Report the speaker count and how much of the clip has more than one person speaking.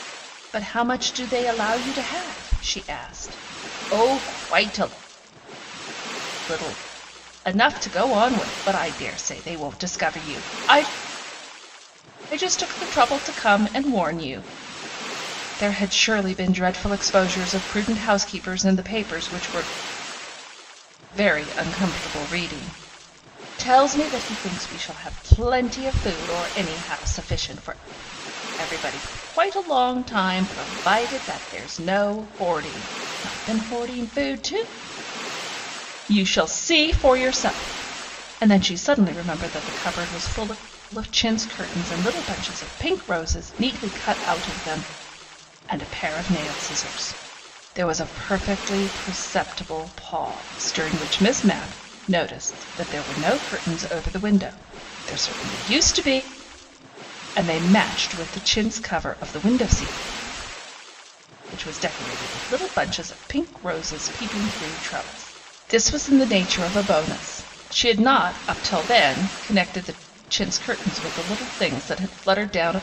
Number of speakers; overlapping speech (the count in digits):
1, no overlap